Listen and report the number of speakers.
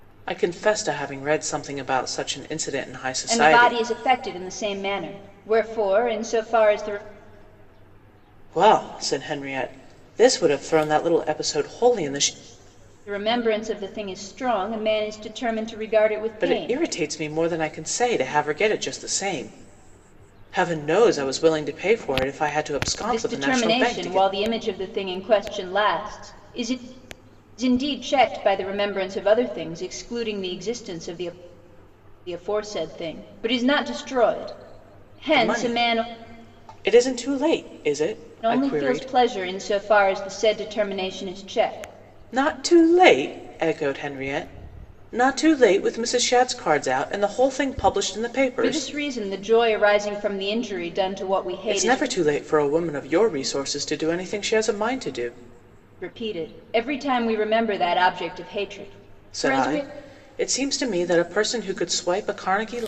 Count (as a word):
two